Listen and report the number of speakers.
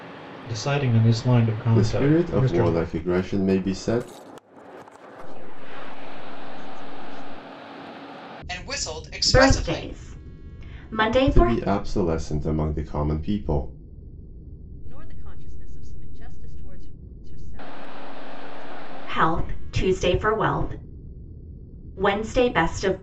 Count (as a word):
five